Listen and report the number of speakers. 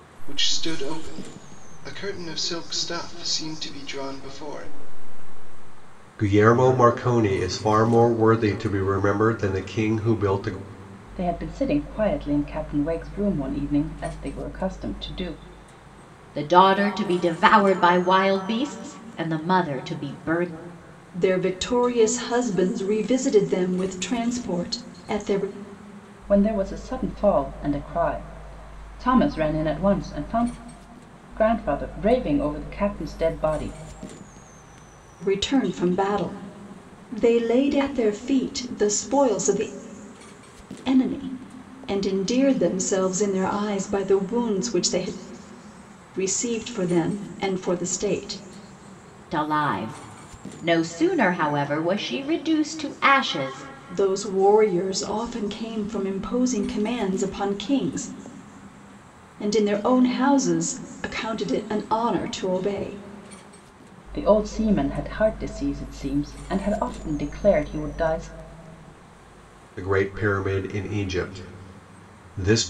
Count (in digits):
5